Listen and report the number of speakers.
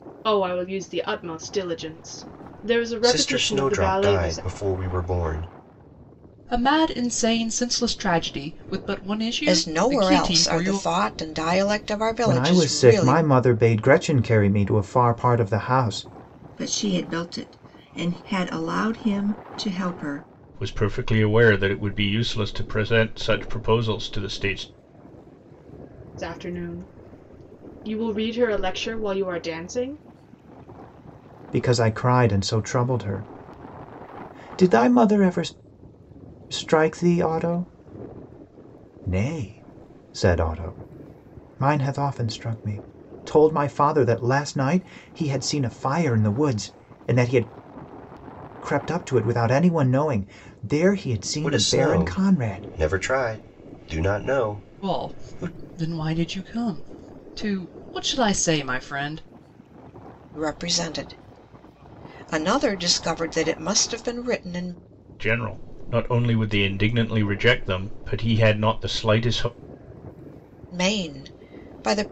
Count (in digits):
7